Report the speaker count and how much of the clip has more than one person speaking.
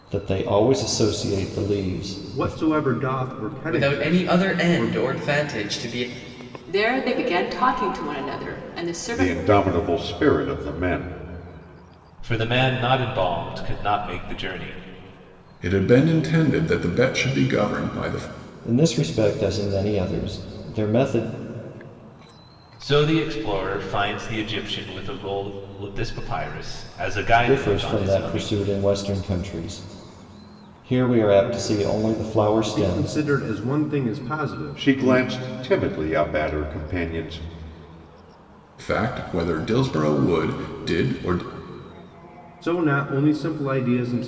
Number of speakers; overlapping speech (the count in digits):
7, about 9%